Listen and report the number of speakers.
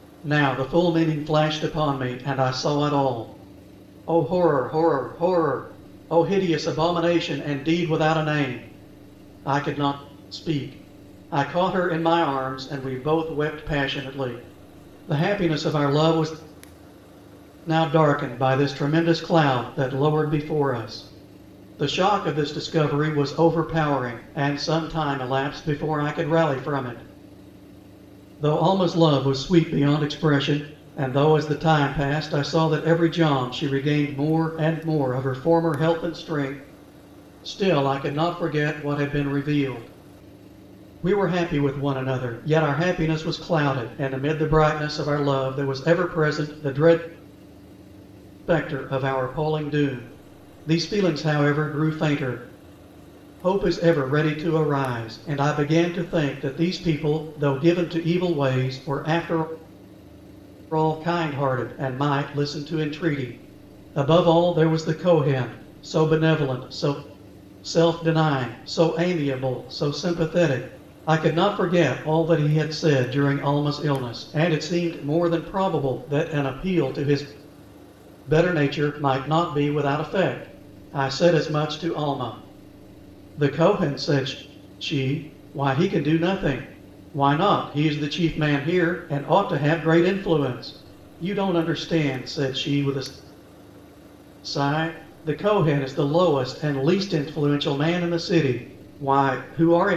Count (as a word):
one